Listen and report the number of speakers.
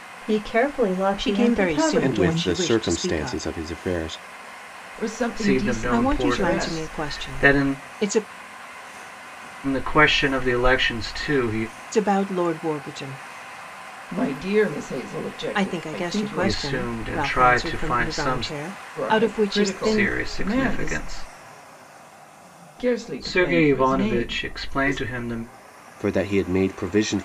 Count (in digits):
5